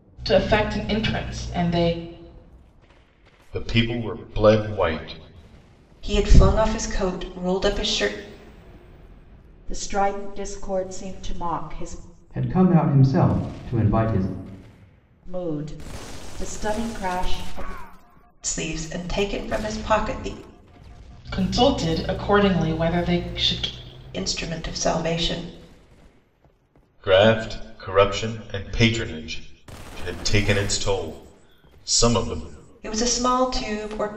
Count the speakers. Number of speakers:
5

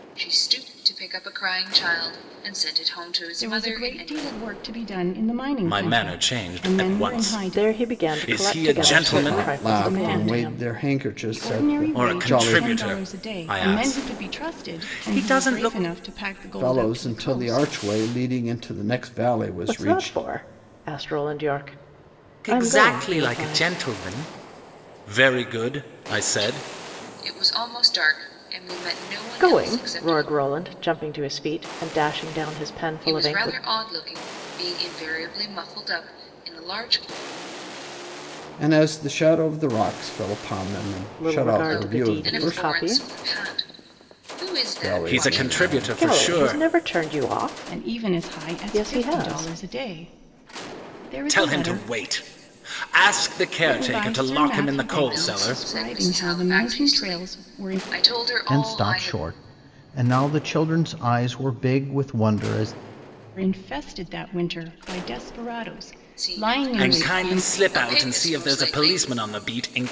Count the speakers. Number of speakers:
5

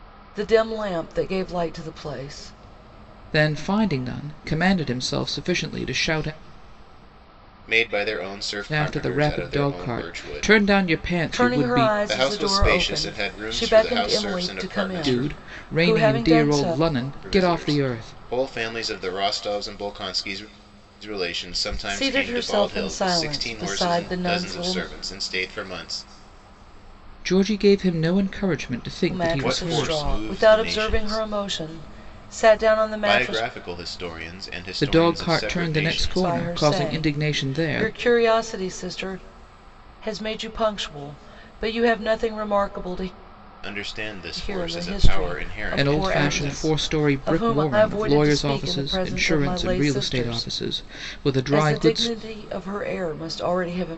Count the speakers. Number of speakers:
3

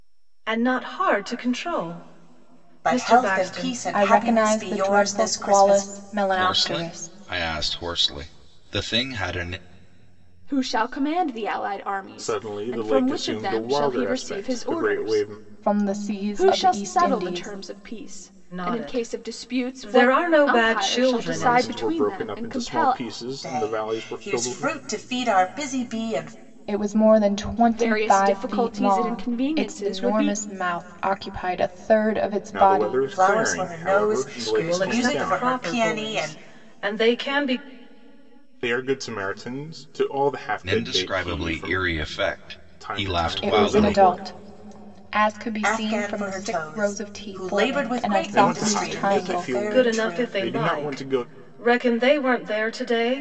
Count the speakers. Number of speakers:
6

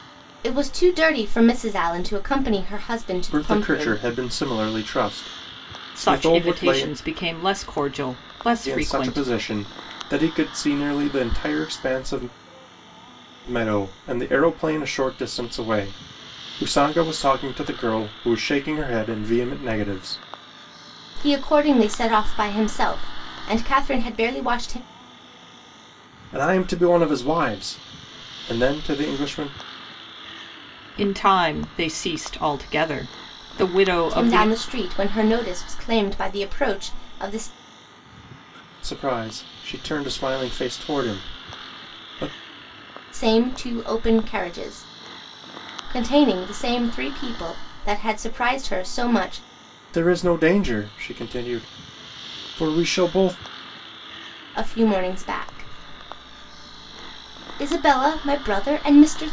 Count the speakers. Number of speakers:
3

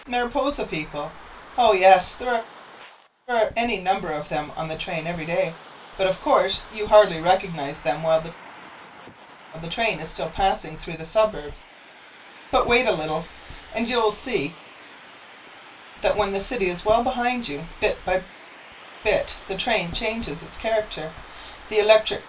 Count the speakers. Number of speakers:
1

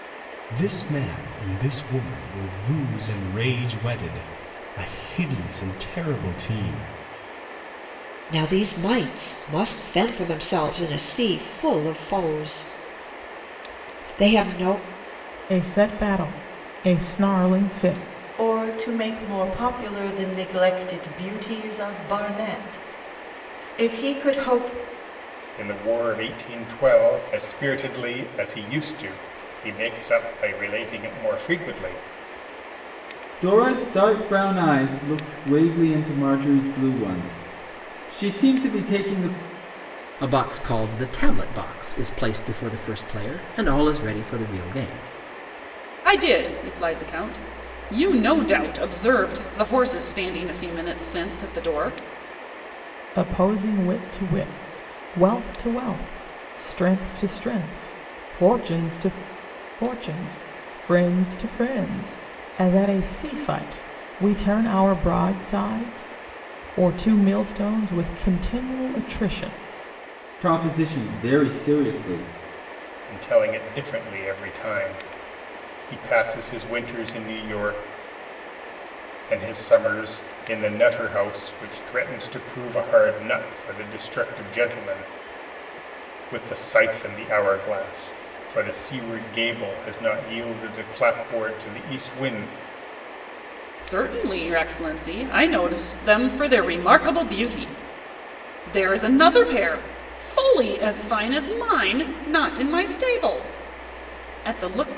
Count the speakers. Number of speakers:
8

